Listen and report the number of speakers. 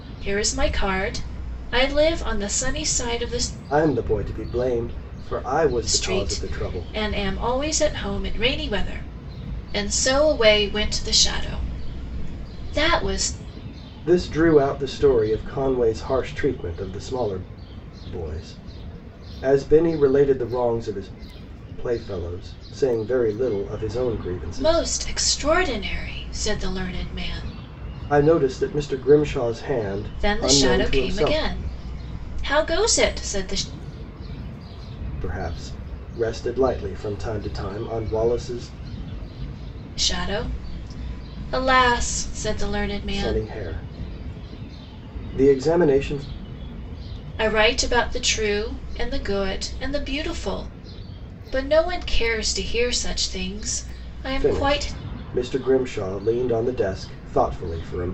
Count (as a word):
two